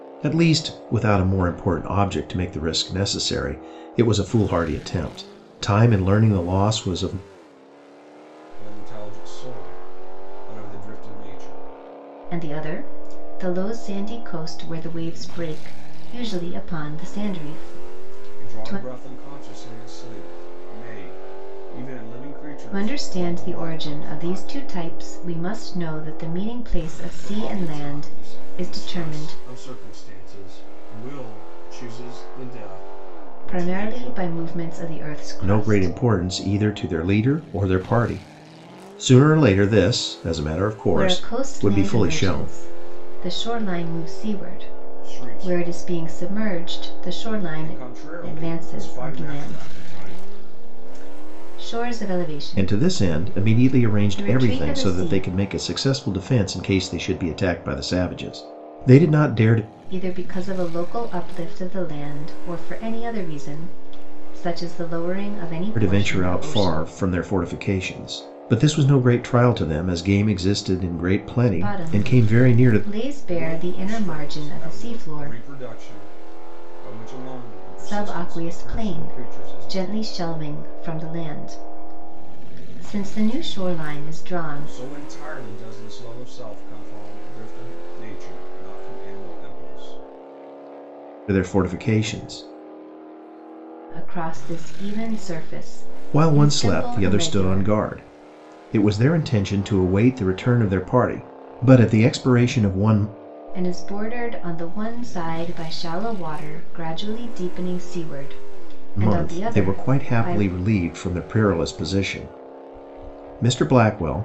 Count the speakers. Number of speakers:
3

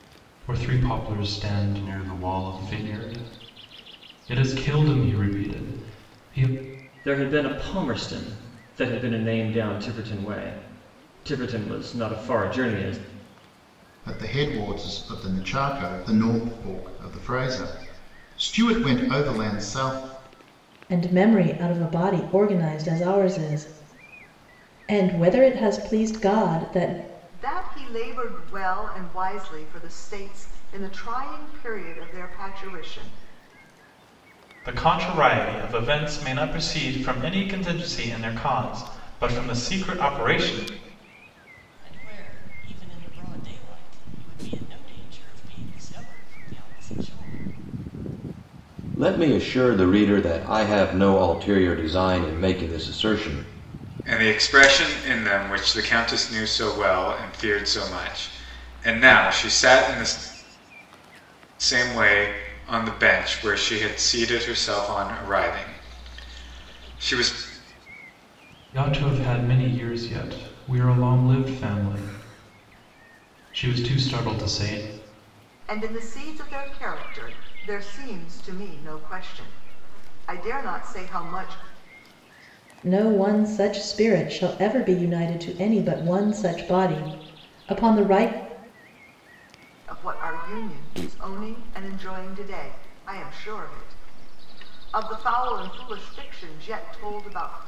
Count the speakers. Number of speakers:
9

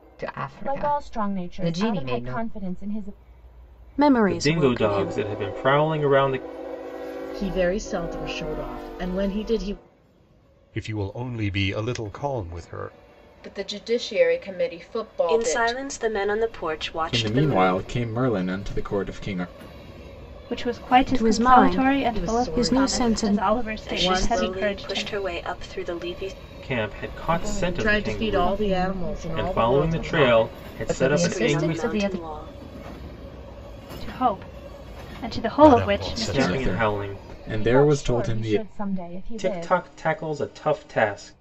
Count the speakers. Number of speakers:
10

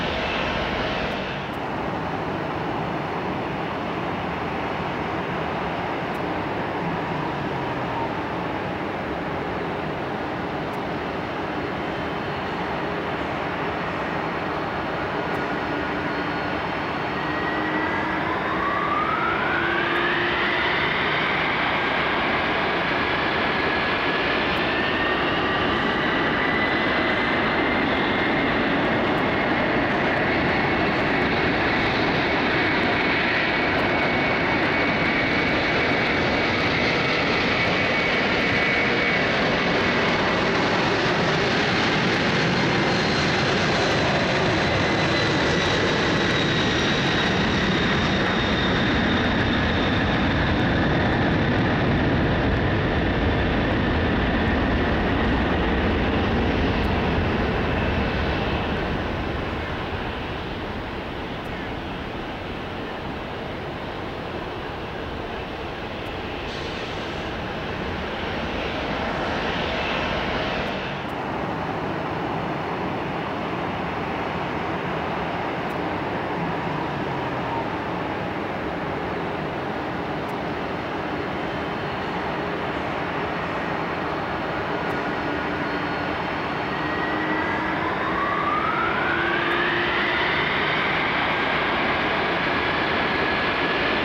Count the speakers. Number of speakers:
0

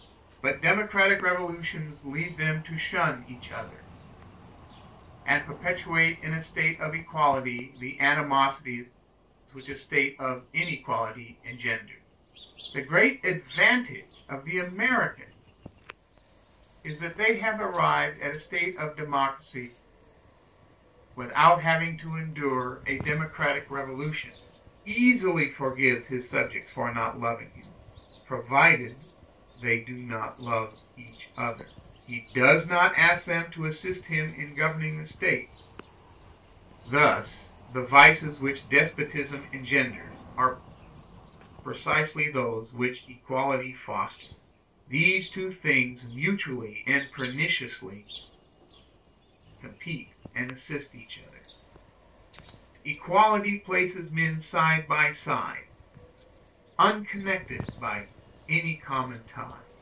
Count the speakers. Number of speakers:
1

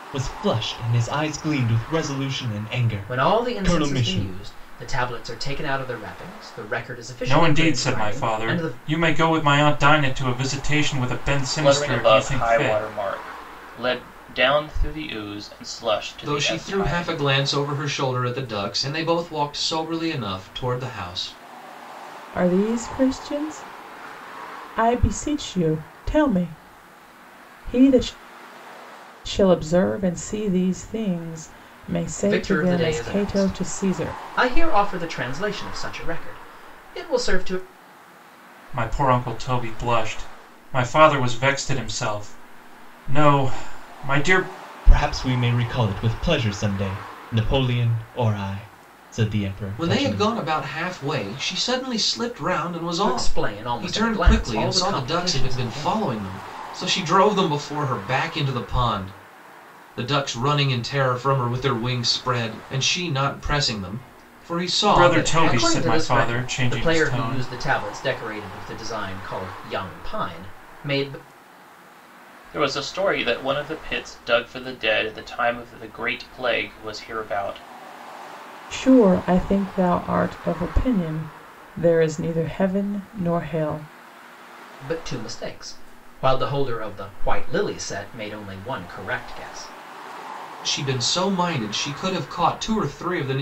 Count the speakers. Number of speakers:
6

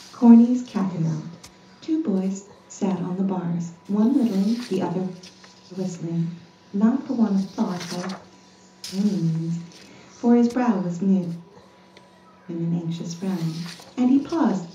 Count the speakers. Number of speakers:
1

